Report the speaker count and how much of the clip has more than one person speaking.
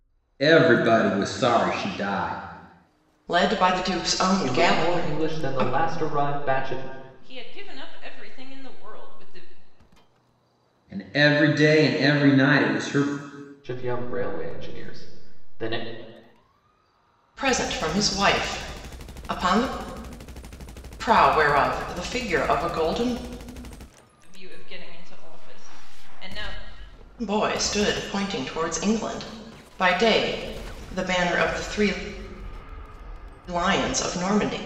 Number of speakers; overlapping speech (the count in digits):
4, about 4%